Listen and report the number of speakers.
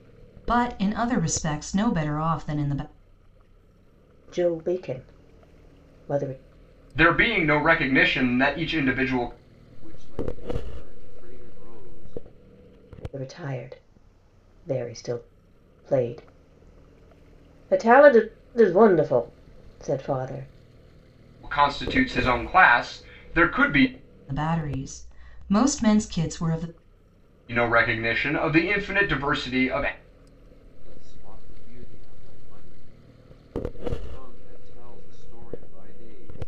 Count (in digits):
4